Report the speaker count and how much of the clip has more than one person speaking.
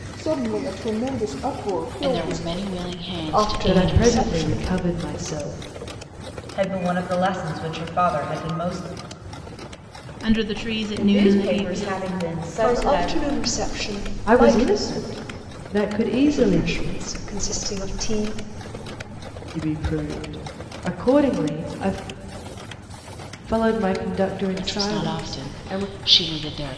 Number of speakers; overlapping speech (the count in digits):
7, about 22%